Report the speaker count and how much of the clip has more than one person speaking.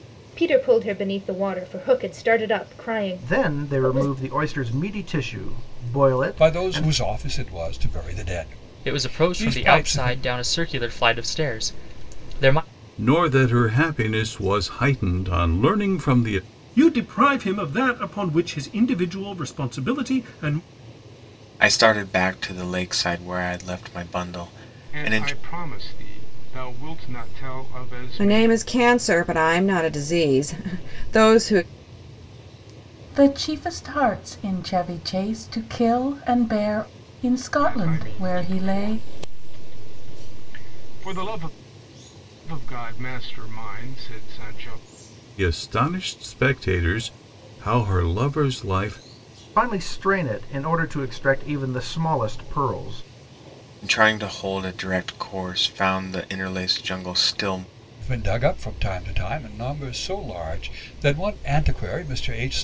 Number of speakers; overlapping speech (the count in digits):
10, about 8%